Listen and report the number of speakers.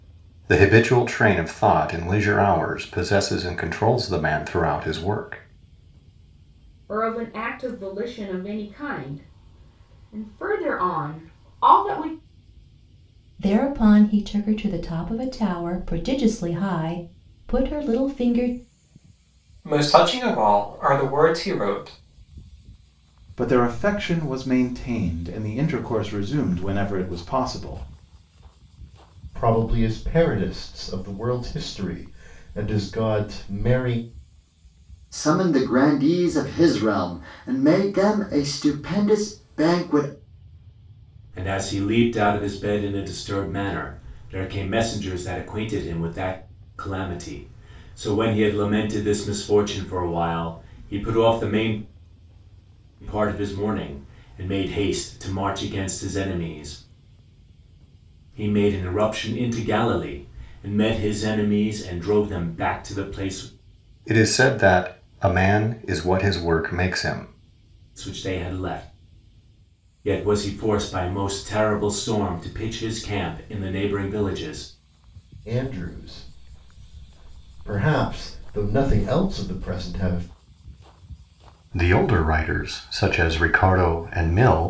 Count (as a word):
eight